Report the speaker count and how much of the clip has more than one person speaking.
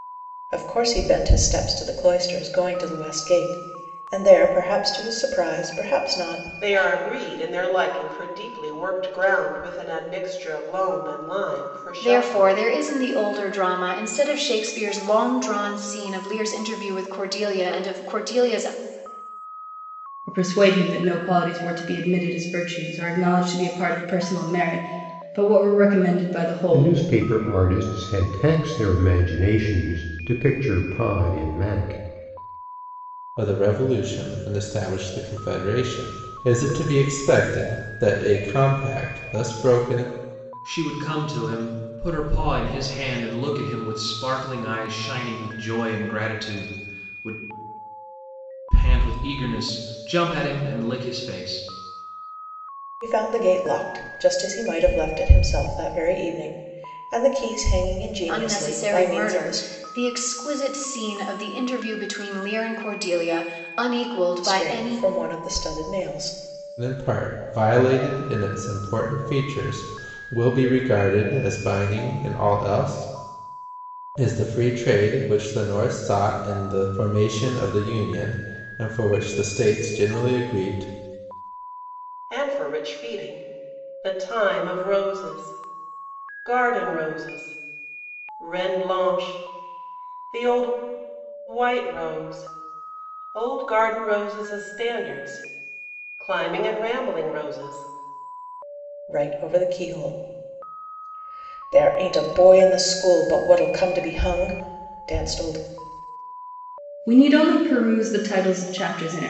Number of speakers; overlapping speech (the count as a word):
seven, about 3%